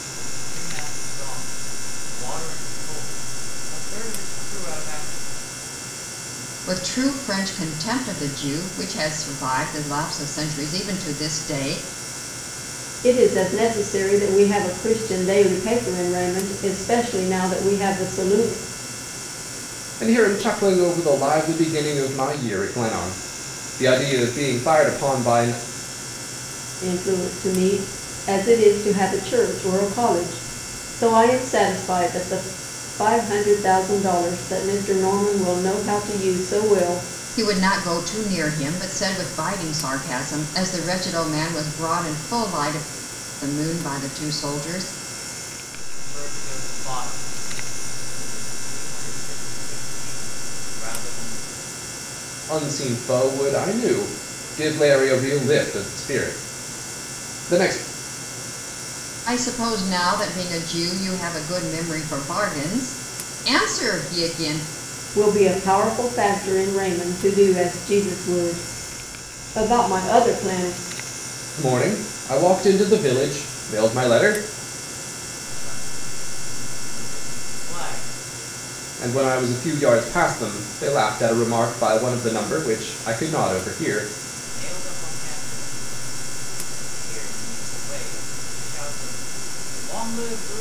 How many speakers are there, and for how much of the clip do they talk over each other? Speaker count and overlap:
4, no overlap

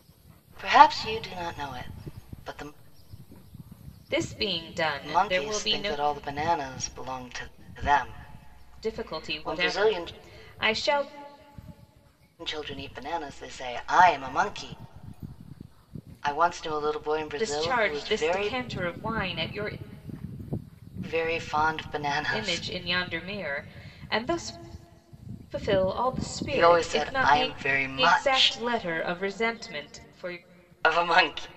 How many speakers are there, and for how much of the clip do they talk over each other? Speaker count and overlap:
2, about 17%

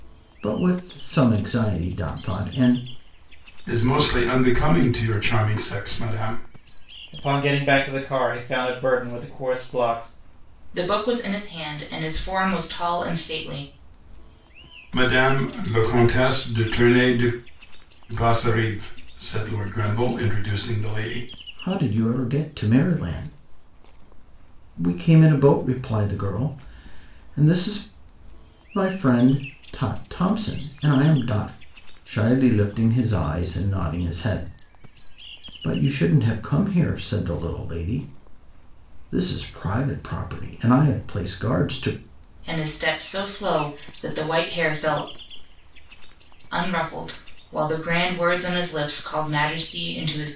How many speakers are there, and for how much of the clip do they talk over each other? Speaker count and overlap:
4, no overlap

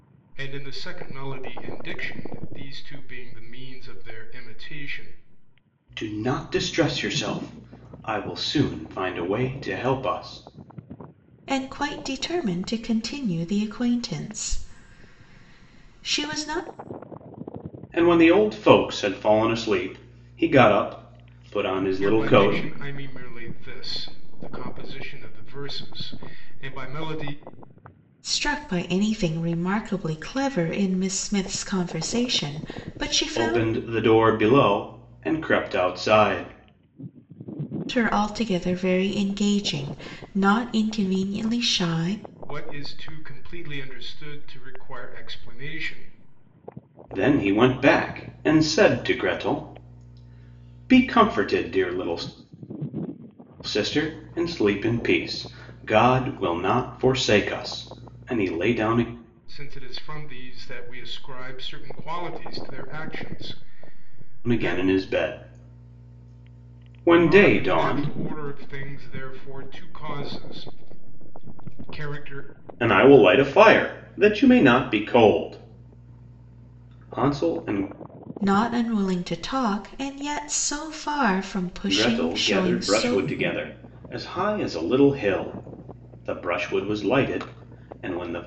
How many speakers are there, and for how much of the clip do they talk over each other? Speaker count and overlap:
3, about 4%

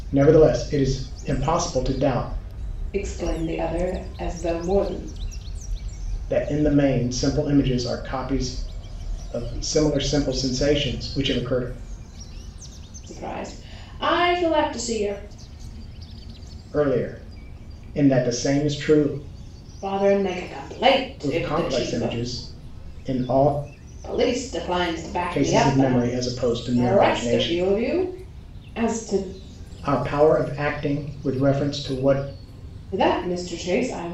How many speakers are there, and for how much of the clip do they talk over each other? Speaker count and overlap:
2, about 8%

